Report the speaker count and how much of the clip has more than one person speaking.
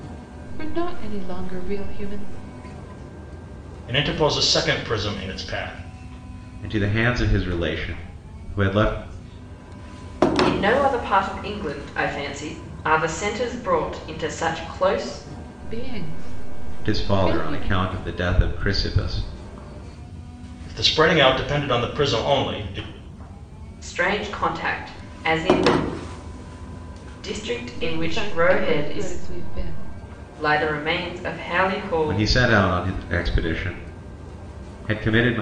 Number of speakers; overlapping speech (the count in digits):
4, about 8%